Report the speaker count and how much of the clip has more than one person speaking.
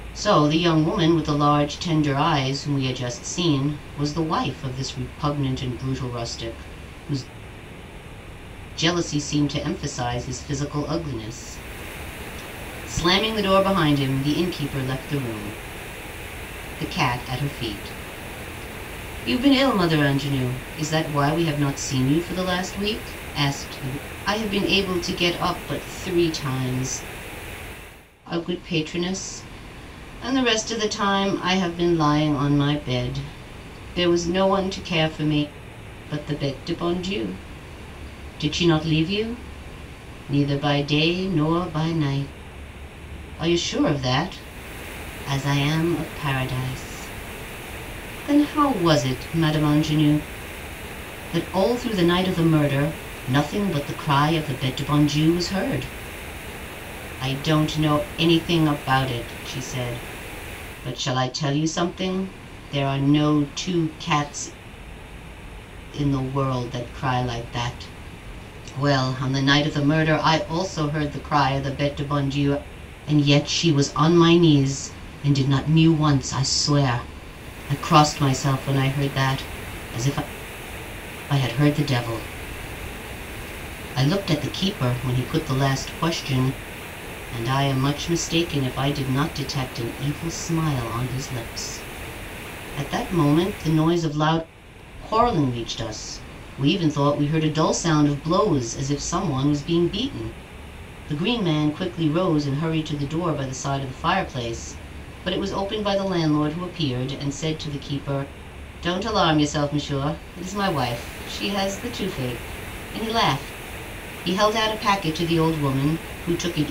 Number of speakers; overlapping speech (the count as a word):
one, no overlap